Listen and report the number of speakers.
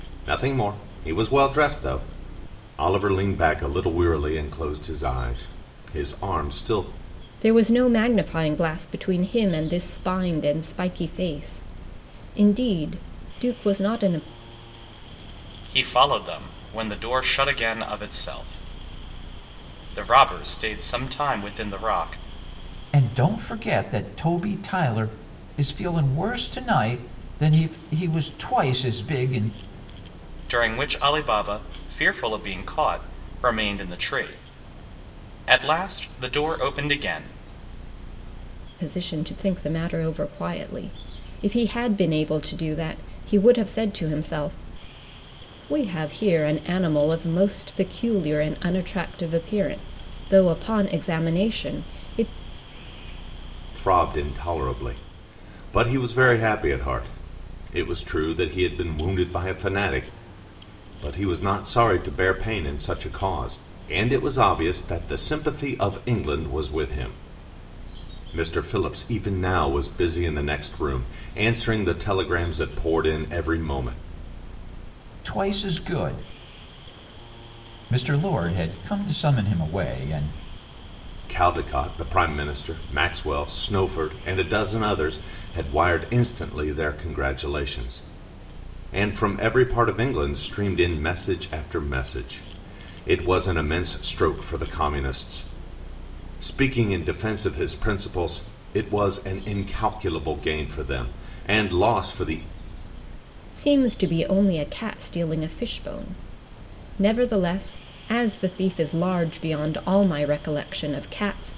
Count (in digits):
4